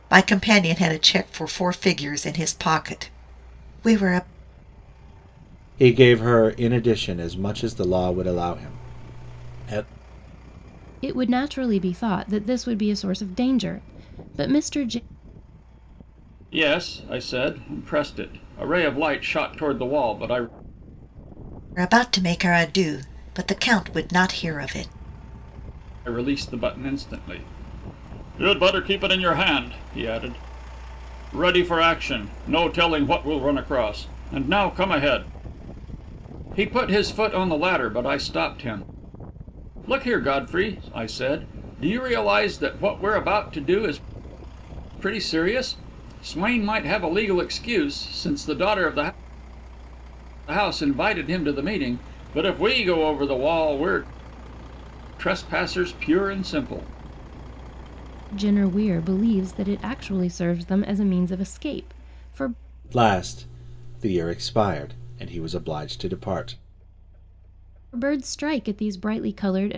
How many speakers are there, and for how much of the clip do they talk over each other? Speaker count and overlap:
four, no overlap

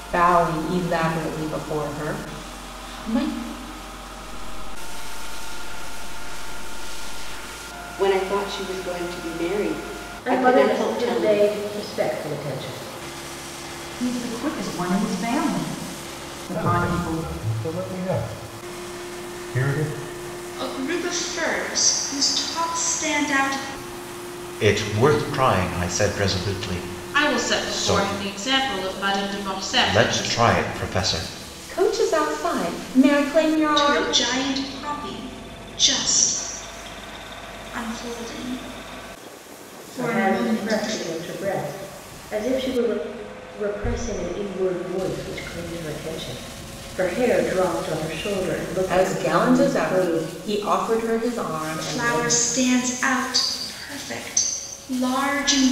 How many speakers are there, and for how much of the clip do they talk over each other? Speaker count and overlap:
nine, about 12%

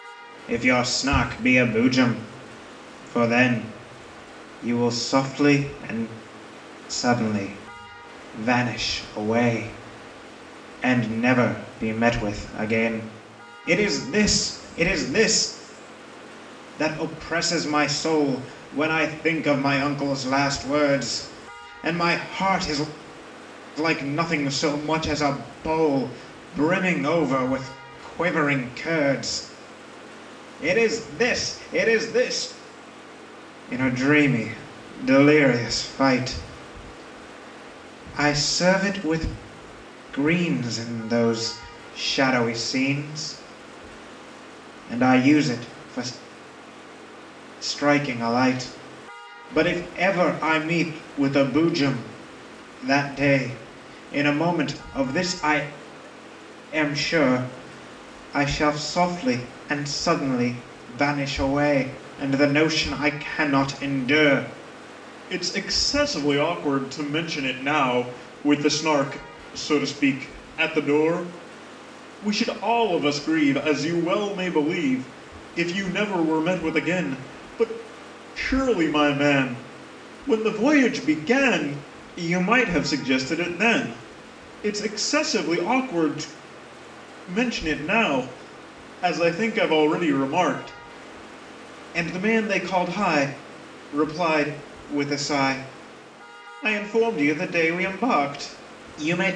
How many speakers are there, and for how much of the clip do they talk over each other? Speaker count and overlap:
one, no overlap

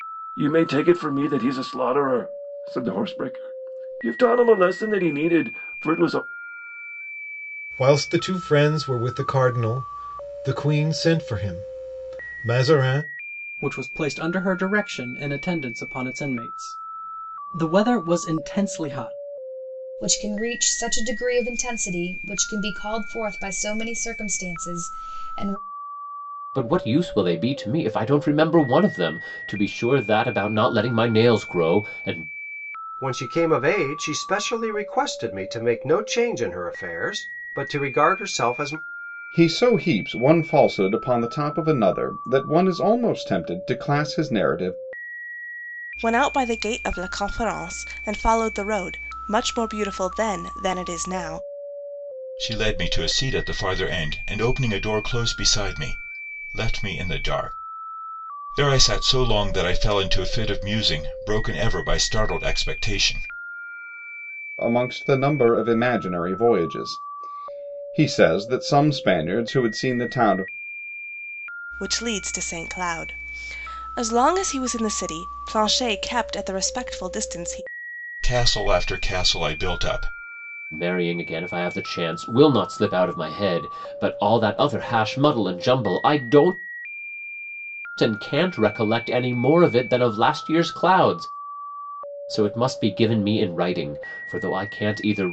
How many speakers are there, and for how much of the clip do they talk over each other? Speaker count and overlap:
nine, no overlap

